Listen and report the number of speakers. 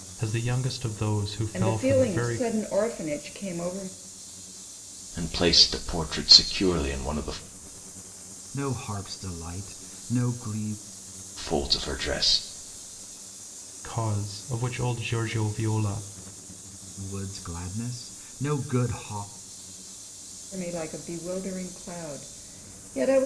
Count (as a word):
four